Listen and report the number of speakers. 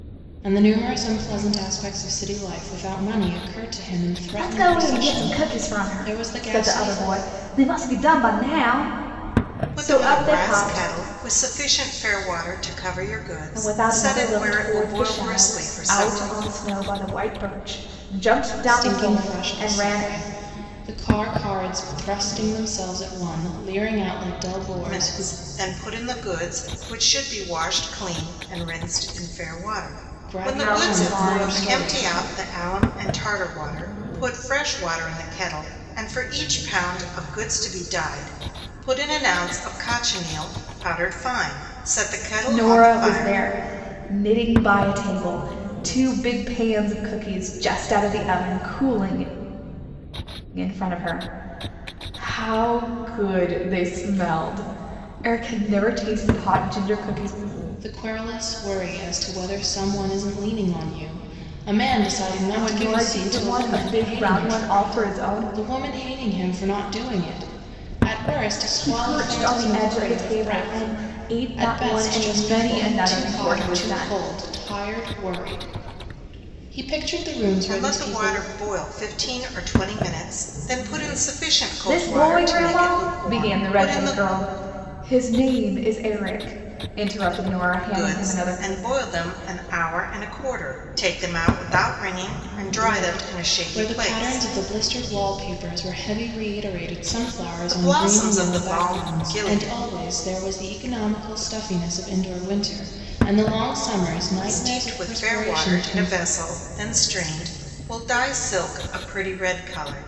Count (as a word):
three